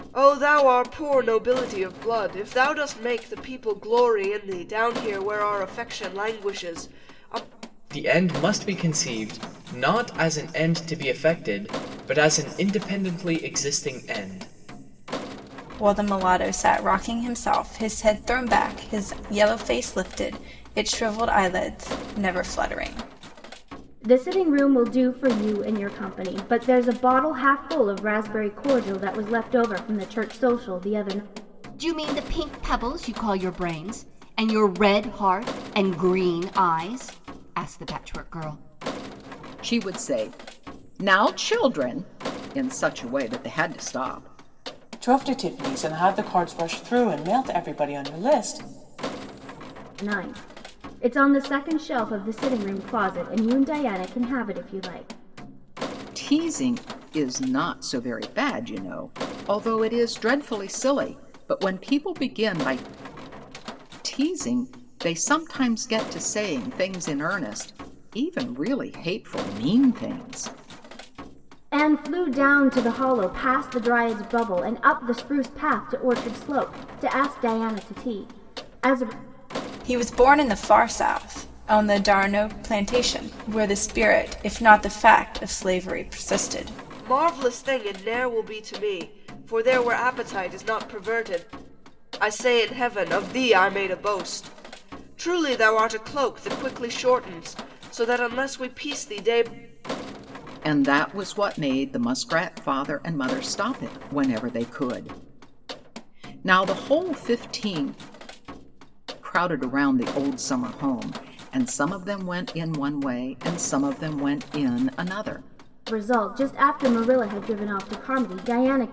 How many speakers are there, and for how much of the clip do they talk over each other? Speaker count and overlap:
7, no overlap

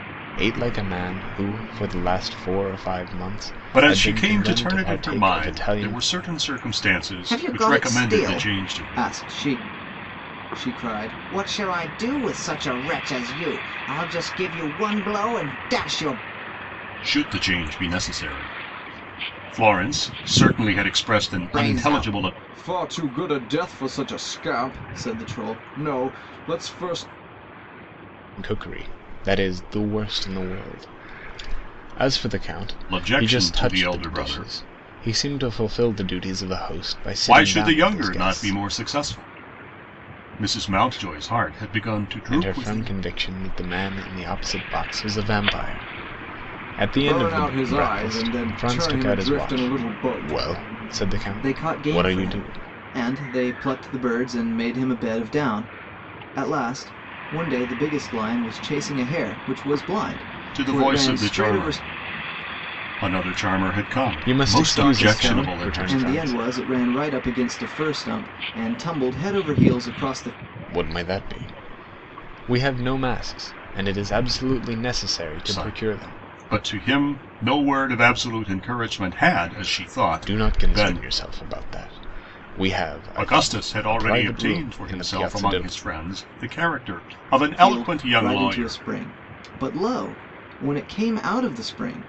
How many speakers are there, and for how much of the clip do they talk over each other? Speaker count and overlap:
3, about 24%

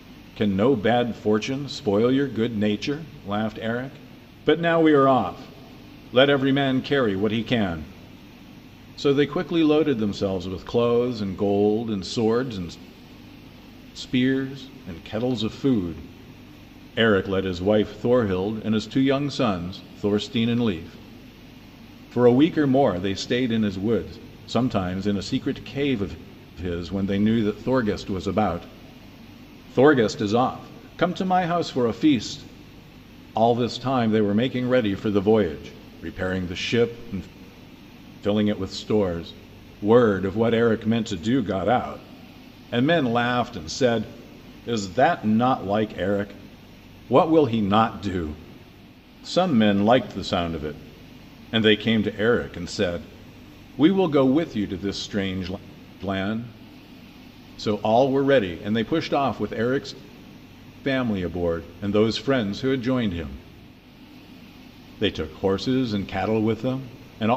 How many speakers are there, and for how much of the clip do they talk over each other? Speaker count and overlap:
1, no overlap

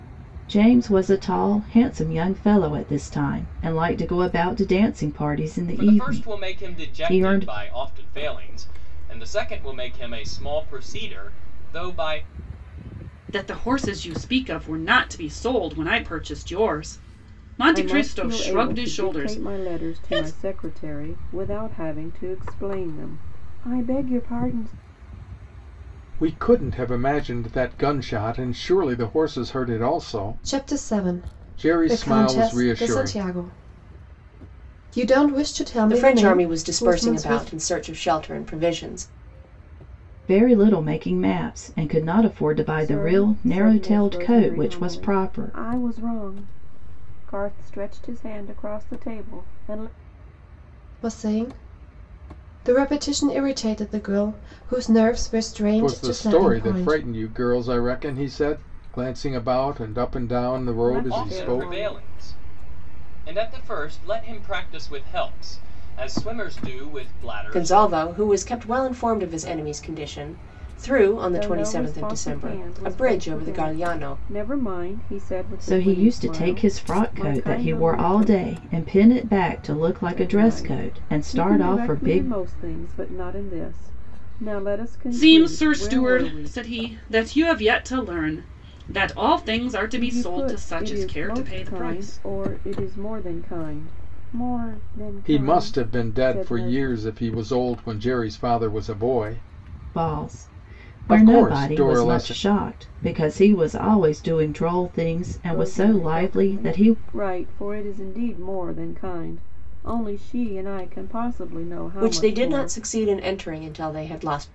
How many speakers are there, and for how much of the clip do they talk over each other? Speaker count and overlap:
7, about 29%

